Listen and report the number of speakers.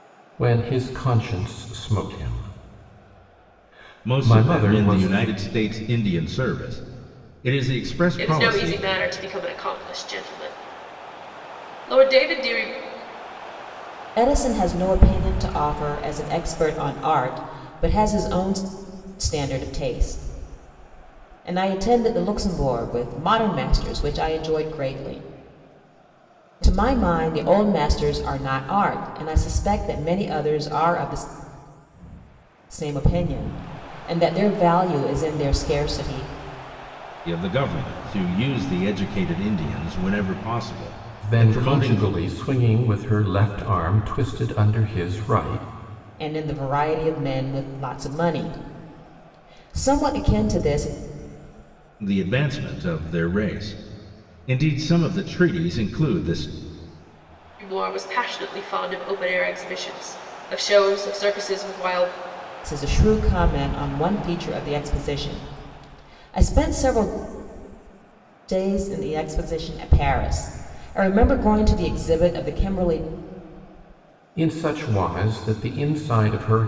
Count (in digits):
4